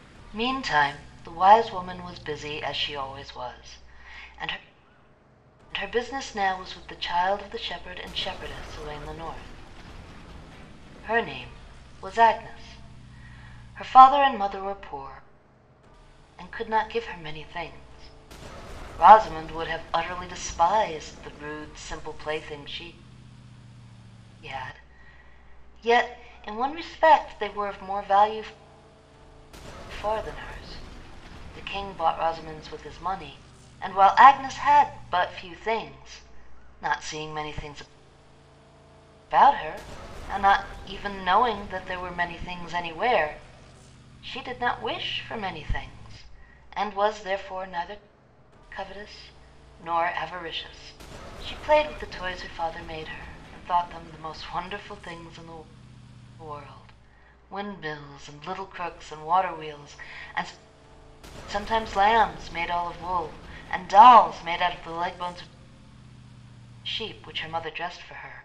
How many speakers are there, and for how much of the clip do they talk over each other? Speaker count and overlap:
one, no overlap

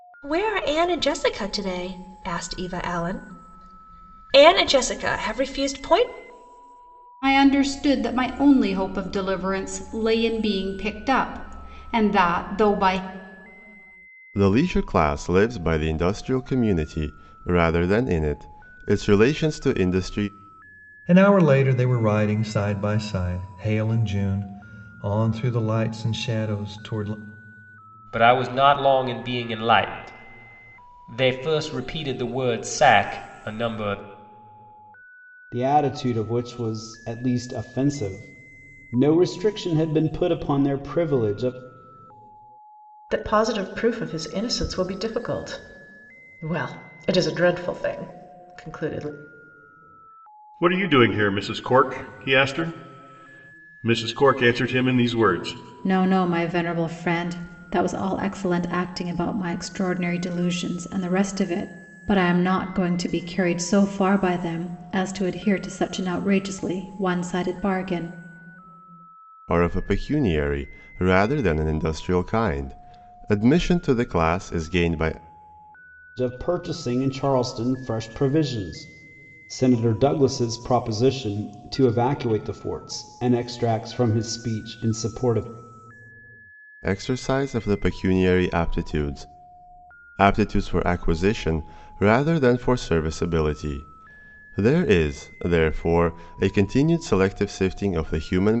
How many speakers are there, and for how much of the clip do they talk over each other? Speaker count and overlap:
nine, no overlap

